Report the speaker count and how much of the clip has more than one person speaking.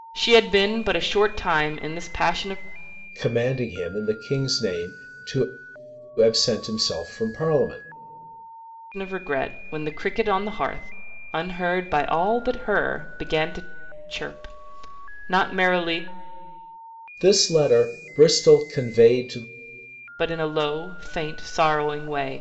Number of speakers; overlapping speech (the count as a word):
two, no overlap